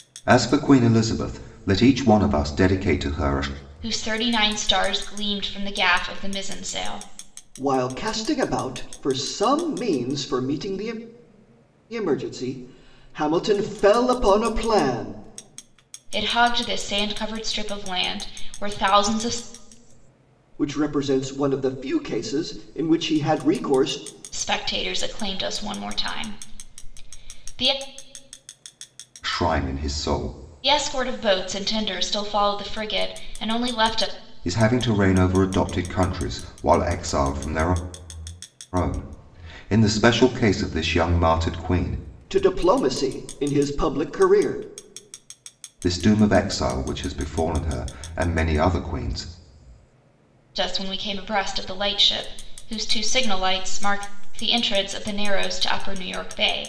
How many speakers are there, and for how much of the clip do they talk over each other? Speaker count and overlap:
3, no overlap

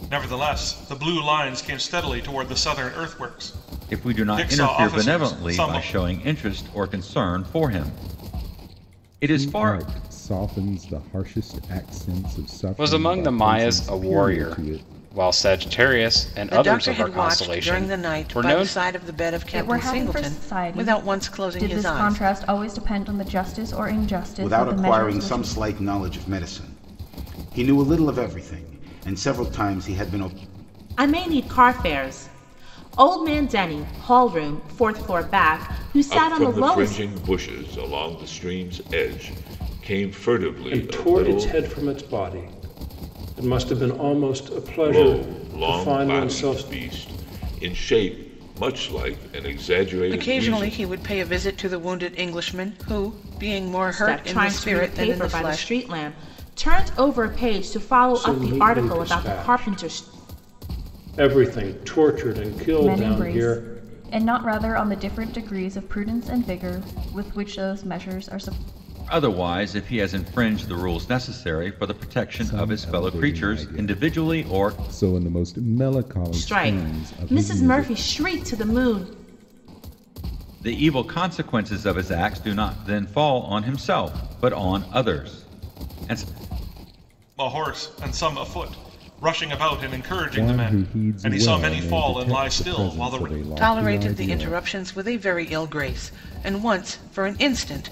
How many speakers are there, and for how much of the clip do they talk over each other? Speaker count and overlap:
10, about 29%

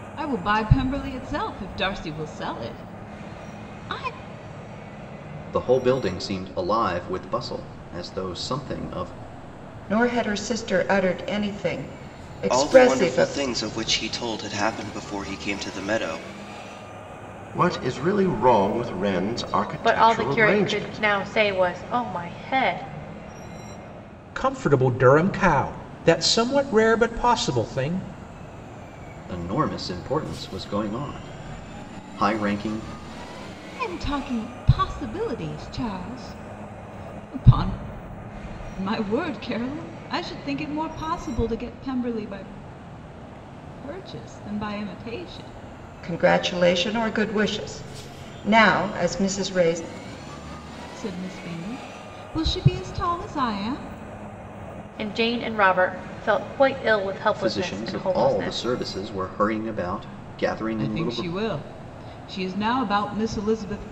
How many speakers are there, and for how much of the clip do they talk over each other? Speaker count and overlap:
7, about 6%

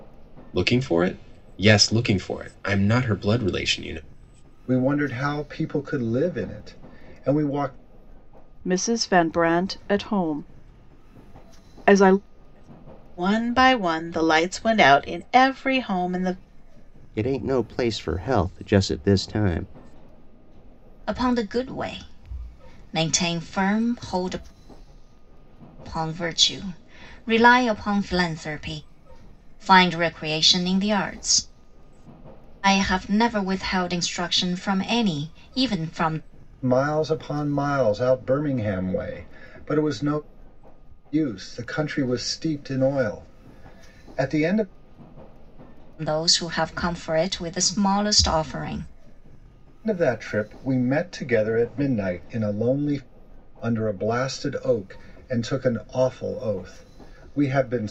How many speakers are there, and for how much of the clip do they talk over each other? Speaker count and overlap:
6, no overlap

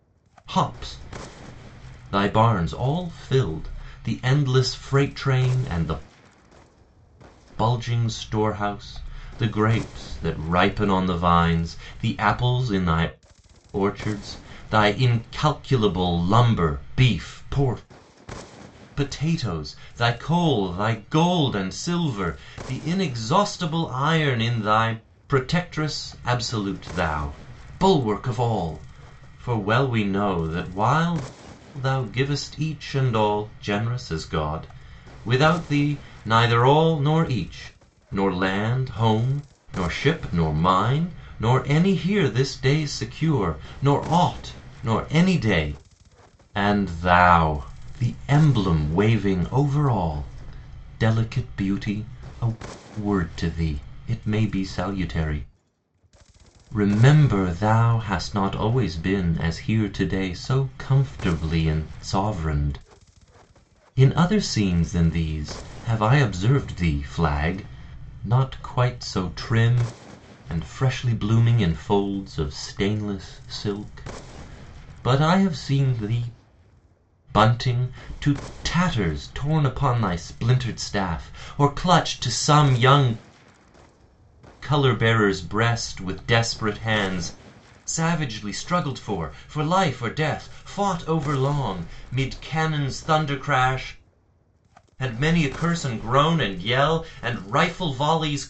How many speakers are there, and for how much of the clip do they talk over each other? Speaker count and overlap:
1, no overlap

